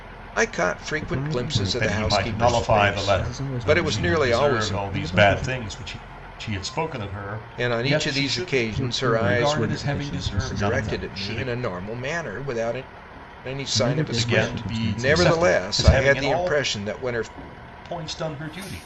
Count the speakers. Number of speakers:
3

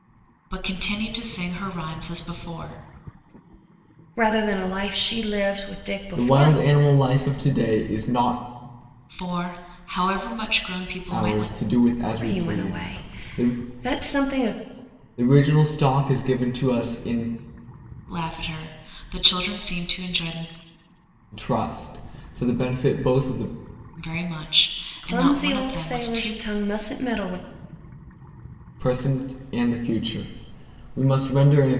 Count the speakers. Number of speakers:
3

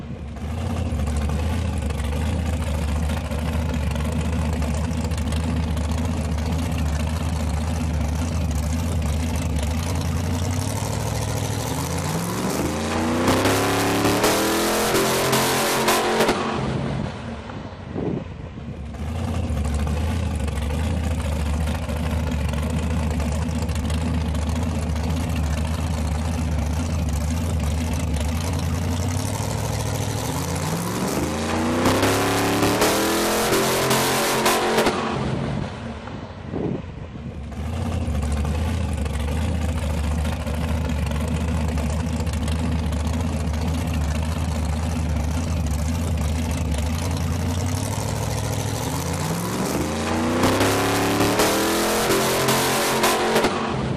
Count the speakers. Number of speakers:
0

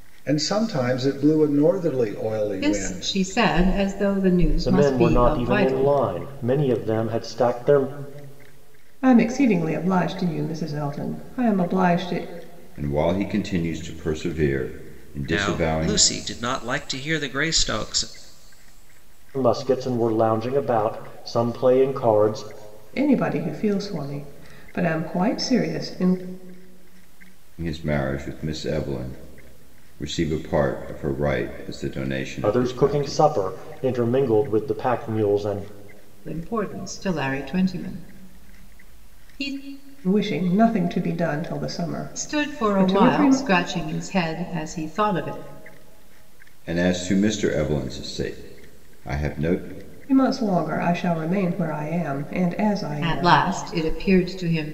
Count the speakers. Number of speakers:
6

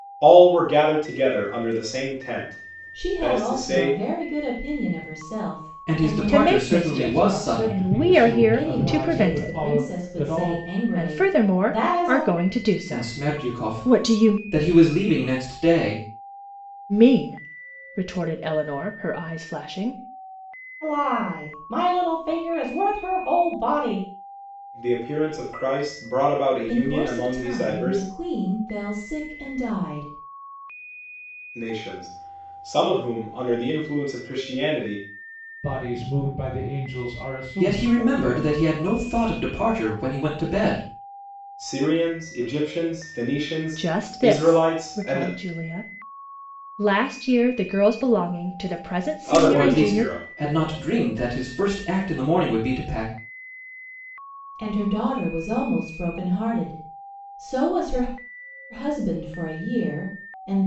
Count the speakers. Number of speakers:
5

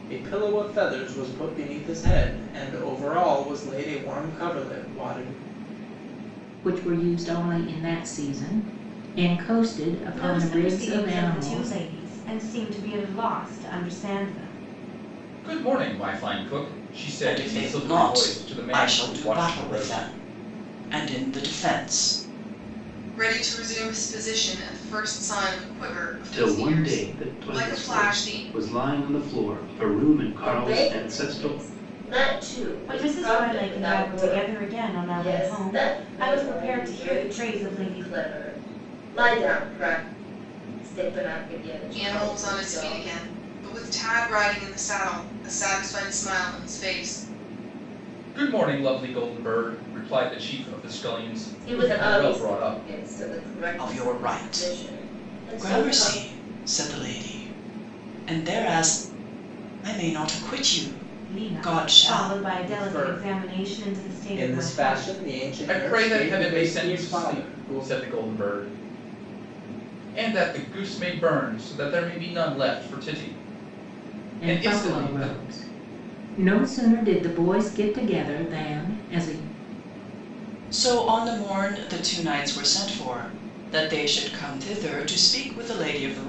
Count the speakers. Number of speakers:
8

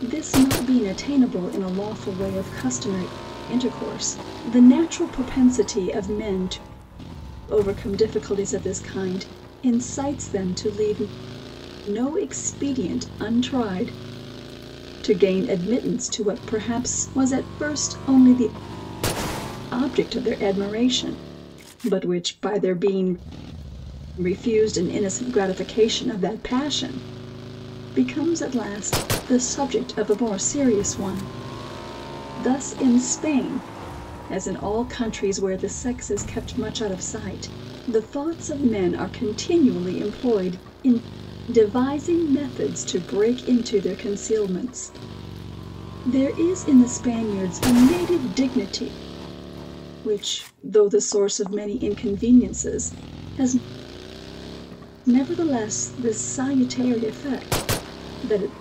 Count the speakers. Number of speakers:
1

